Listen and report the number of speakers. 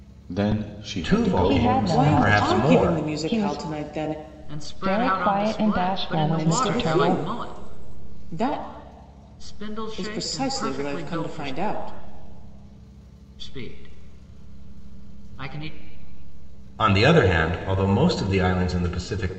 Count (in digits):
5